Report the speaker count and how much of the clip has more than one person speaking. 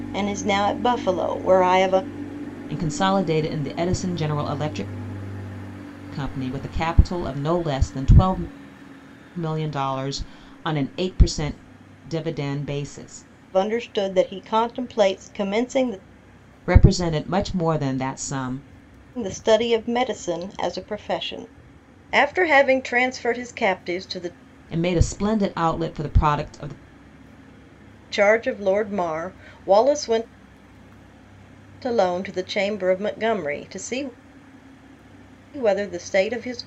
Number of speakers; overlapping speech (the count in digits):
2, no overlap